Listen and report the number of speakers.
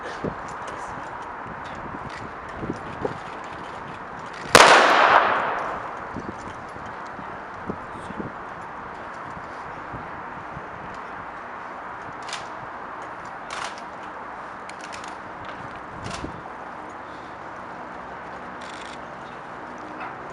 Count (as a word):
zero